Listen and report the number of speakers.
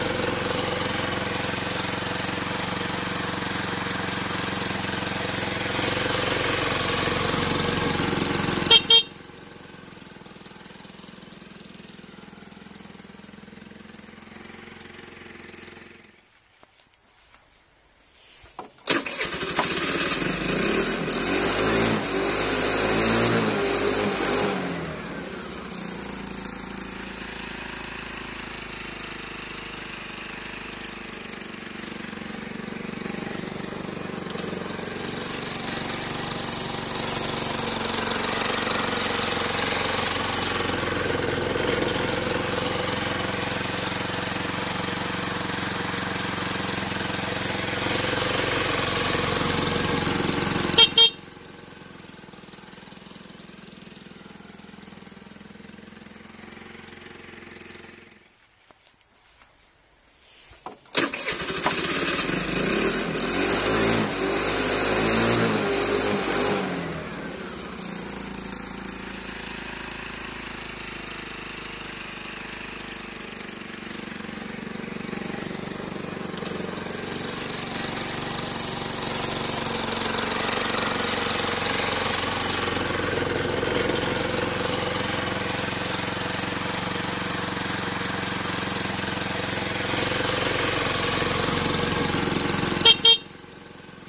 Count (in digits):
0